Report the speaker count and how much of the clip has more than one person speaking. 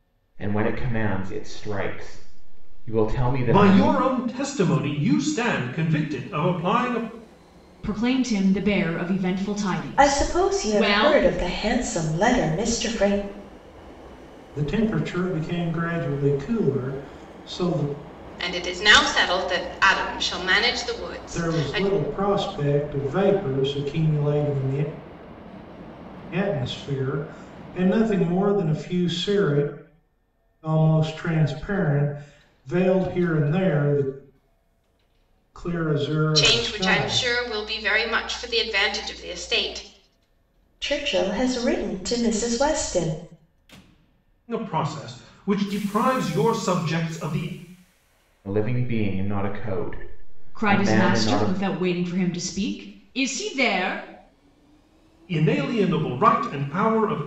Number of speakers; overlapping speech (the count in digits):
6, about 7%